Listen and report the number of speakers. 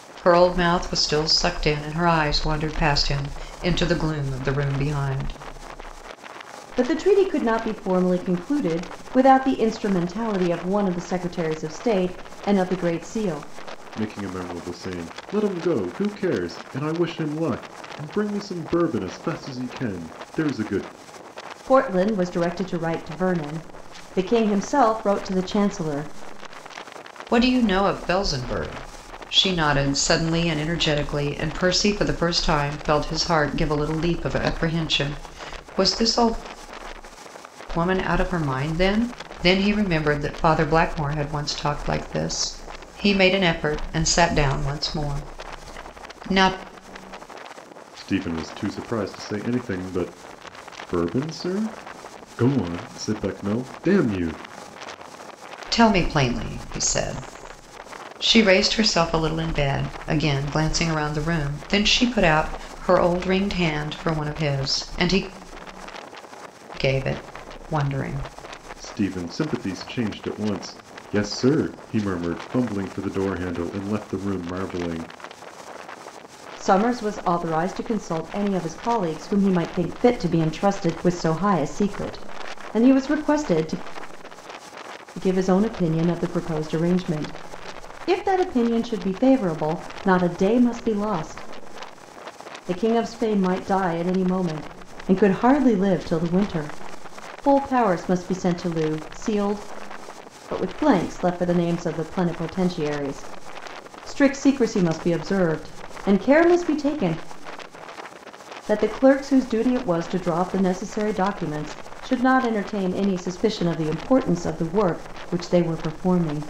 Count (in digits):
3